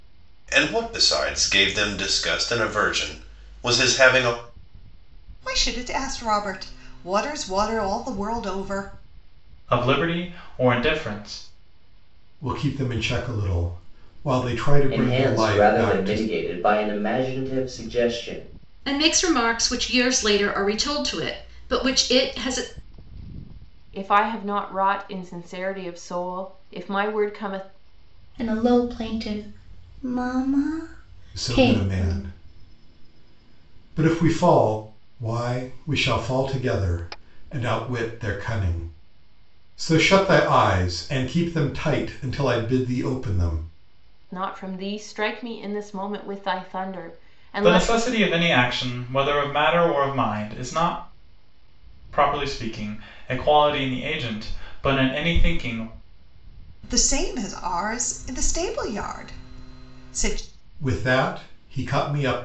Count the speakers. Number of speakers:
eight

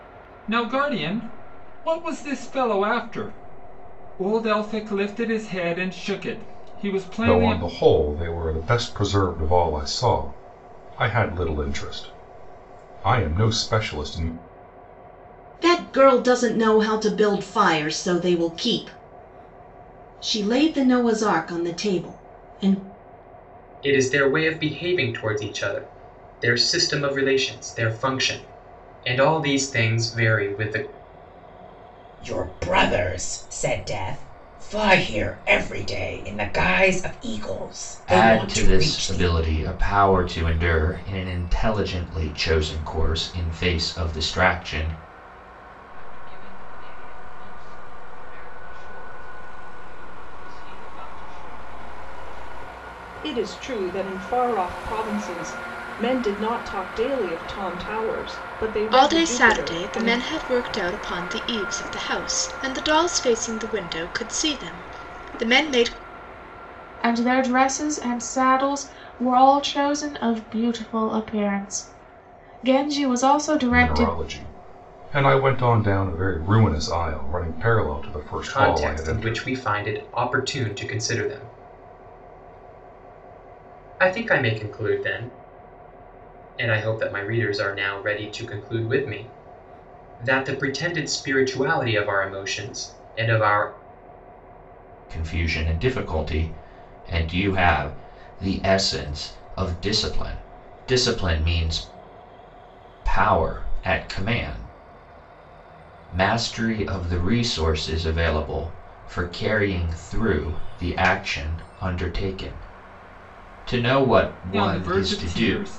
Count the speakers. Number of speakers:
ten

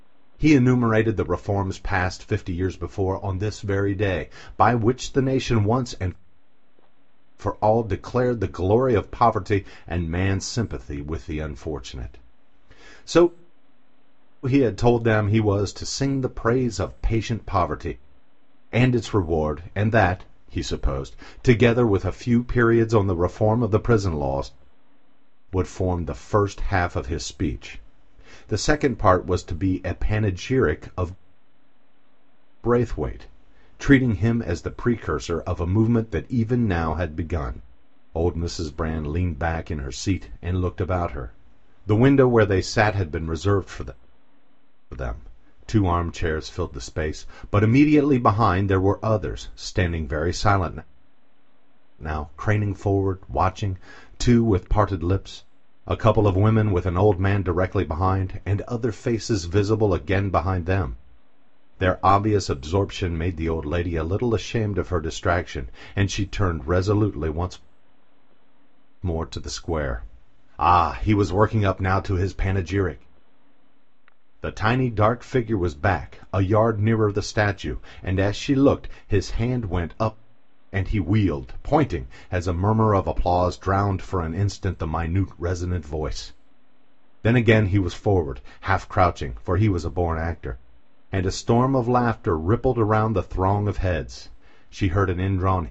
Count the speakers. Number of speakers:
one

